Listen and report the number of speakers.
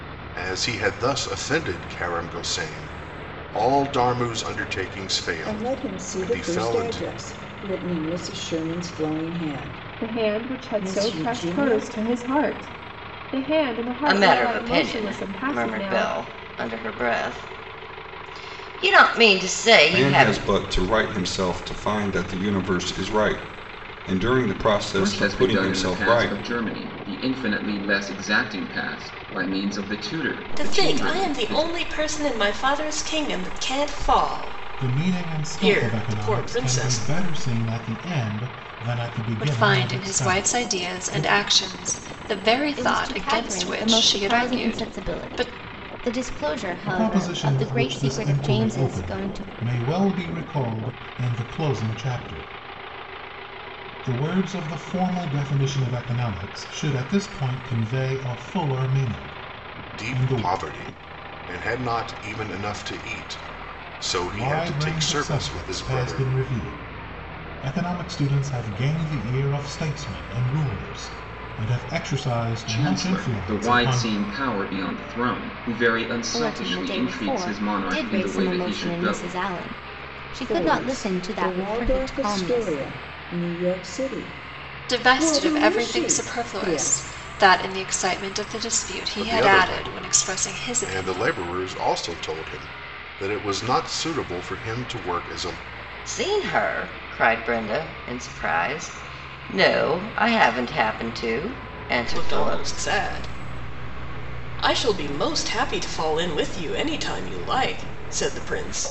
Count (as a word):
ten